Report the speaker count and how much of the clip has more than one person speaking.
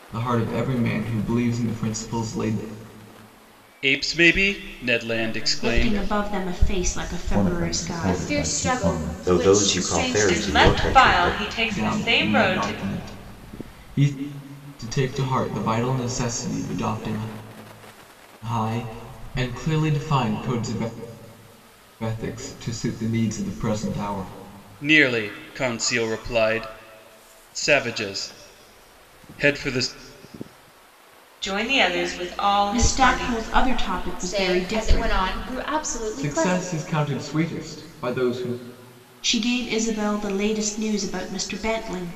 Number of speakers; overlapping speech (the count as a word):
eight, about 22%